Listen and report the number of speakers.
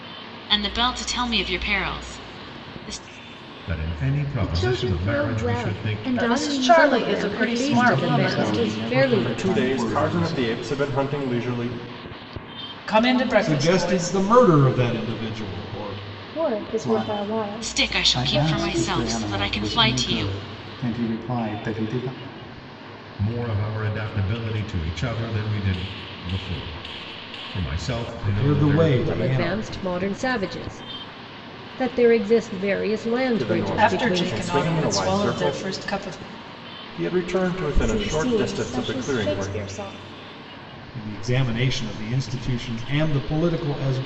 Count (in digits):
10